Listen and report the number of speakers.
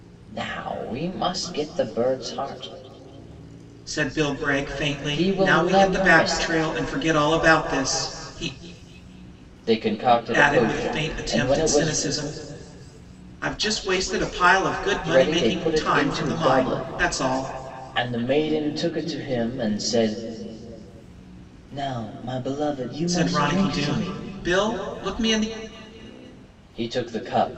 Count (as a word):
two